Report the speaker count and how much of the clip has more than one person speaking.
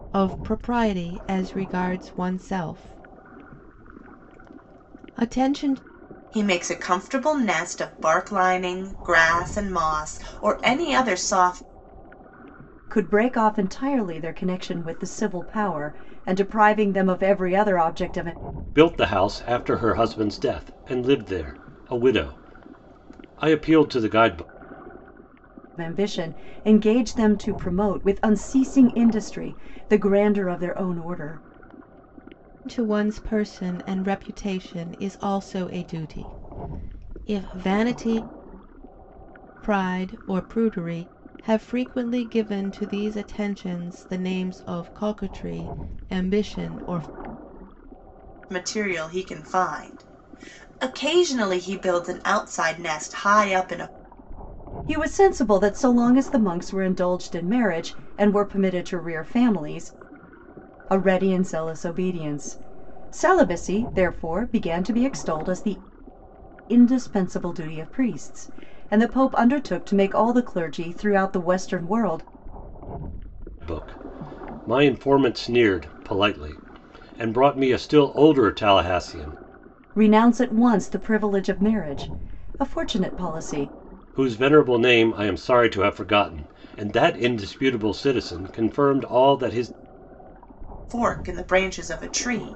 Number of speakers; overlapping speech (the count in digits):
4, no overlap